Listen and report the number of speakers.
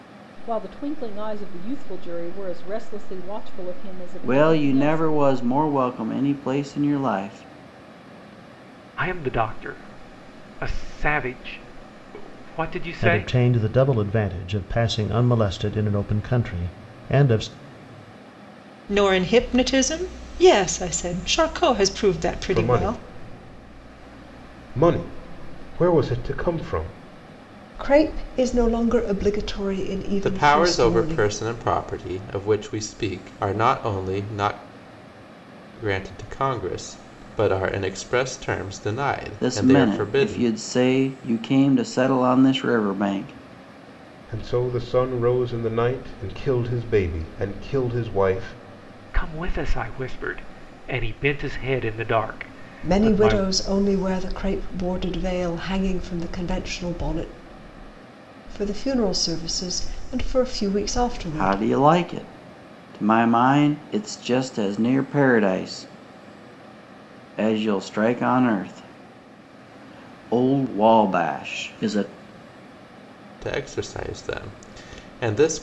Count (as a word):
eight